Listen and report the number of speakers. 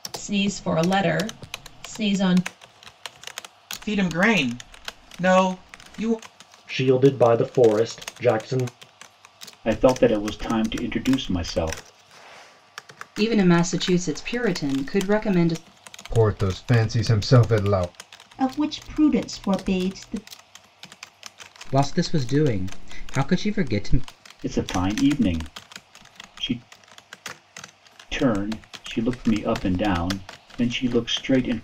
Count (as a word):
eight